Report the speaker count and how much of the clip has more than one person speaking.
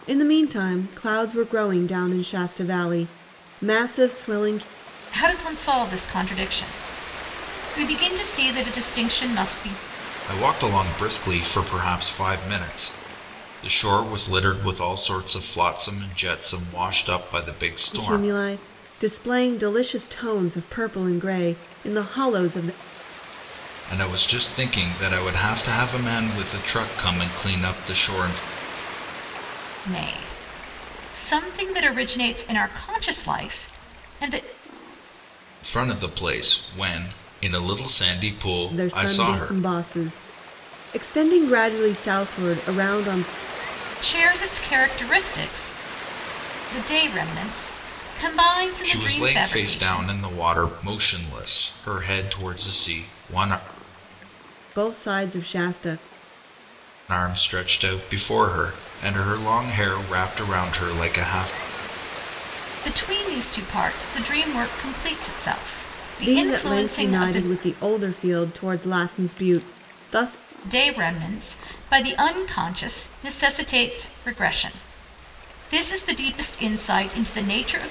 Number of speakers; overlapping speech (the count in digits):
3, about 5%